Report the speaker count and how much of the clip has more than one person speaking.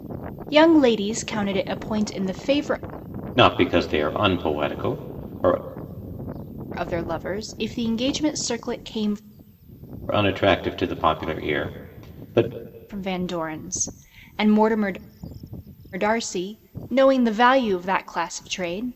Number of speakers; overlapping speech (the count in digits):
2, no overlap